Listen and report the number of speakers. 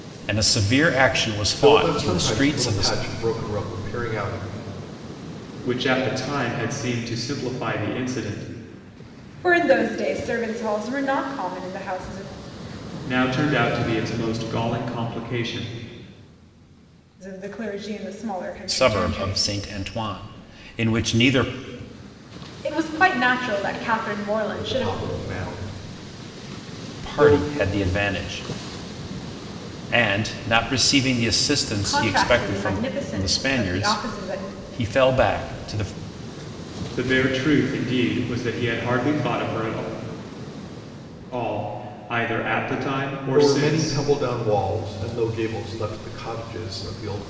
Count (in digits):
4